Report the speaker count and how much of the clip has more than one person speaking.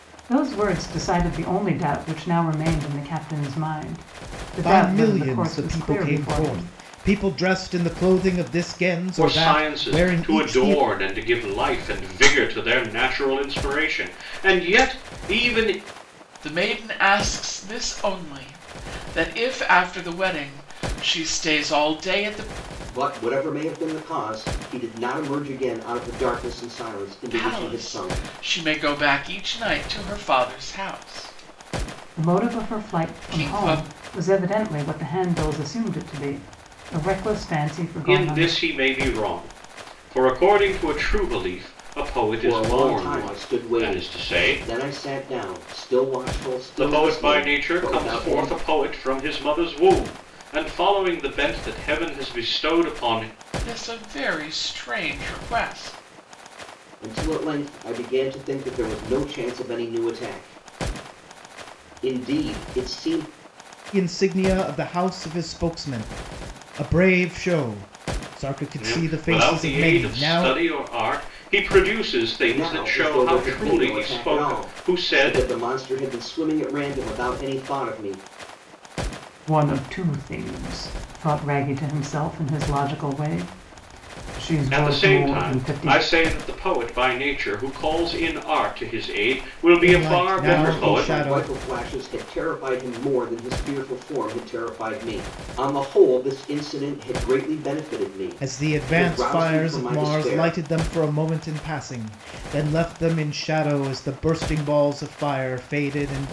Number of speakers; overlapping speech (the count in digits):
5, about 20%